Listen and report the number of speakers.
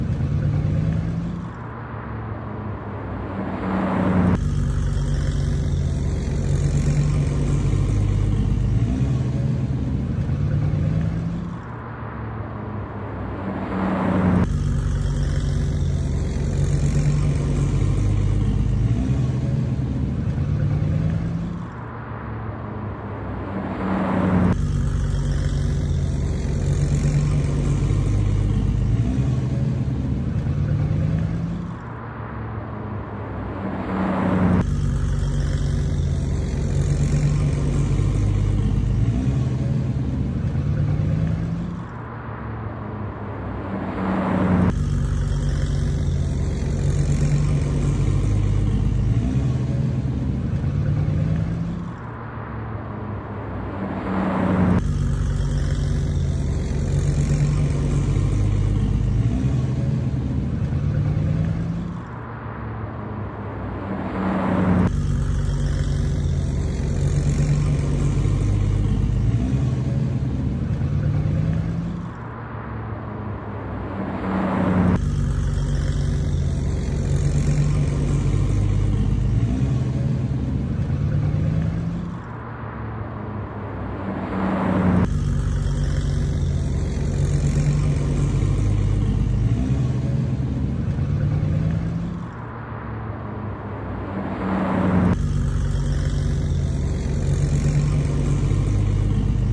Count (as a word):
zero